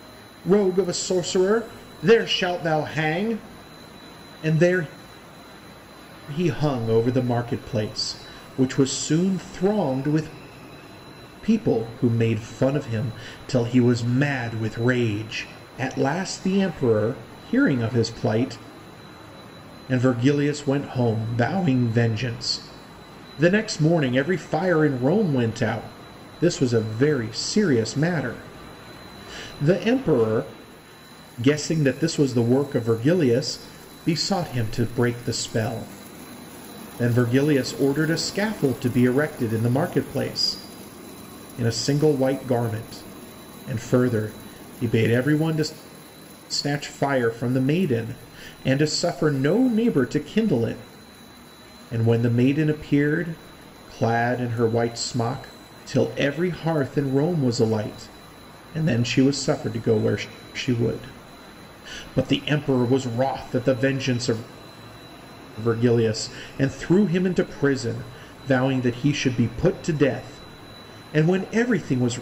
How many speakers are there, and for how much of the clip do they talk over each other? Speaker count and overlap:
1, no overlap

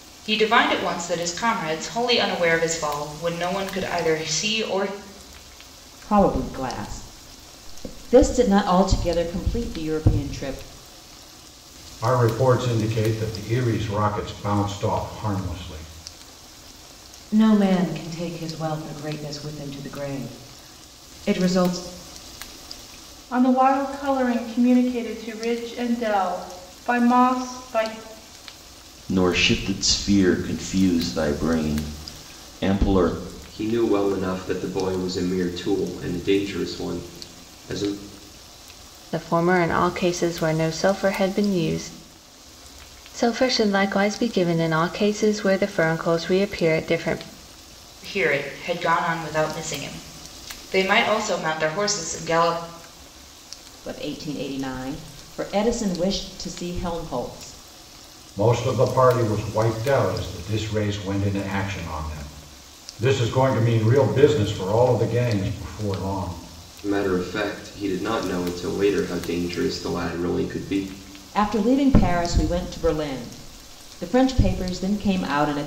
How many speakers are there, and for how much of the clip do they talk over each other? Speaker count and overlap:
8, no overlap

